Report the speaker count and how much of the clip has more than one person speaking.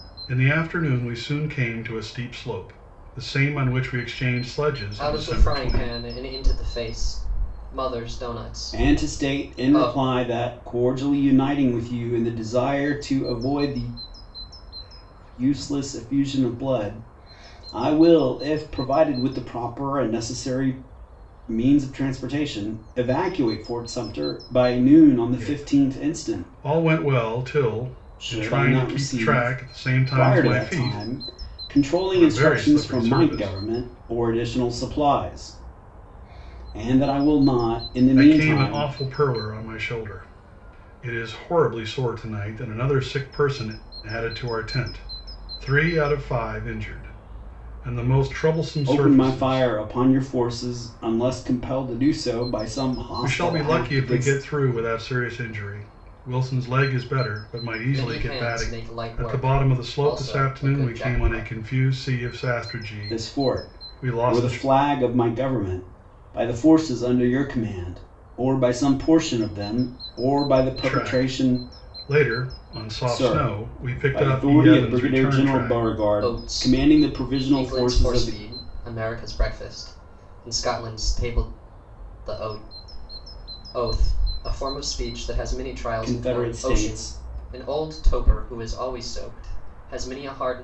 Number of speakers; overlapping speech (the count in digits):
3, about 25%